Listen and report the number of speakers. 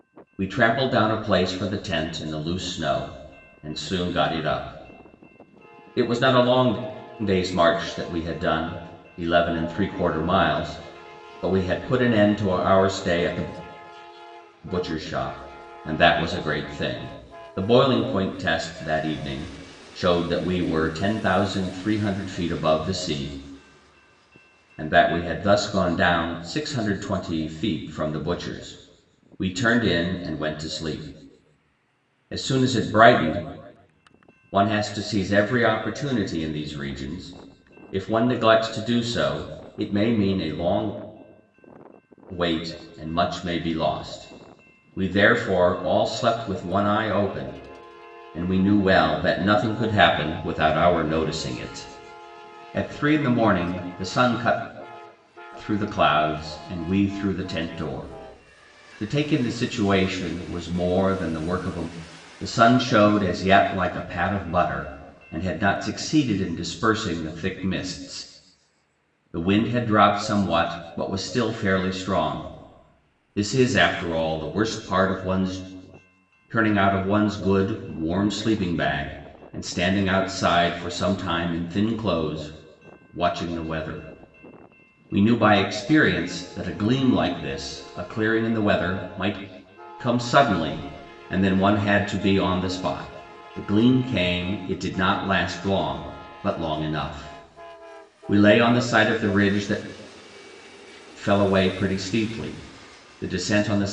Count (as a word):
one